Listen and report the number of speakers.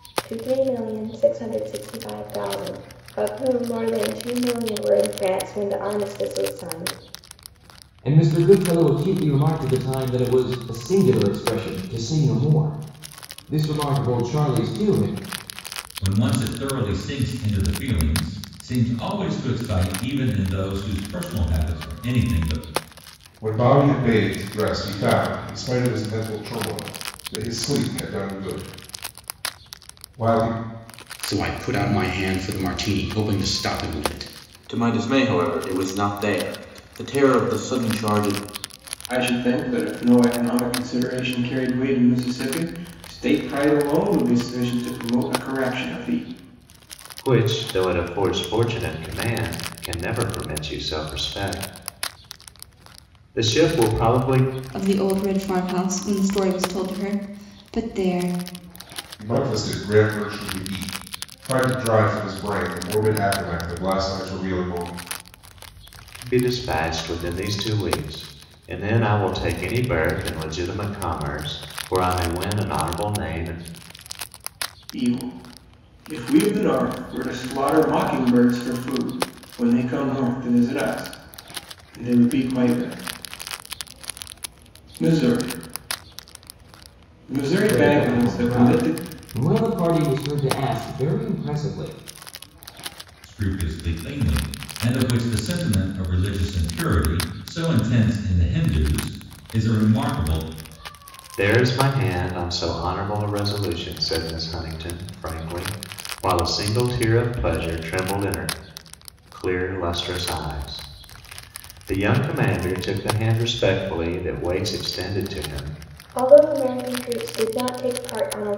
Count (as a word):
eight